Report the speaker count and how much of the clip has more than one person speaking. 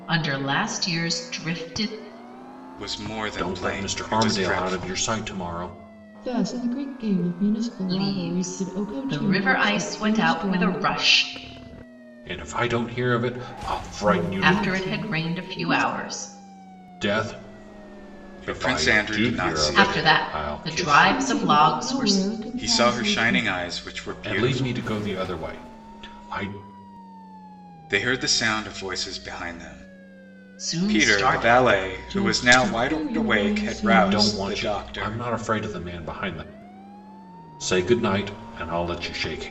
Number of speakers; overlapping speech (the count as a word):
four, about 39%